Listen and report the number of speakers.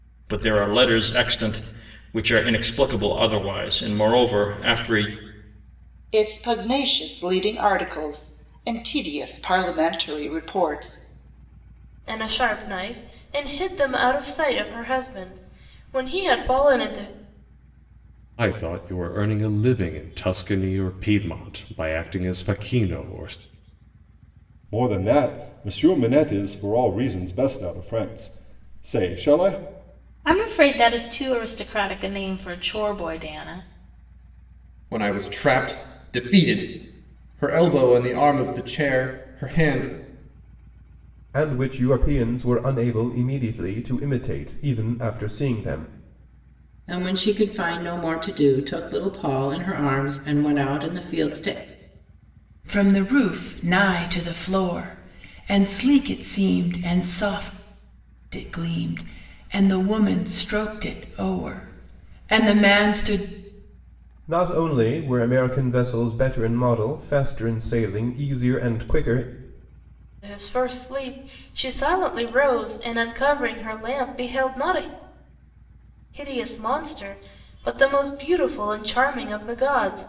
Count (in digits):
10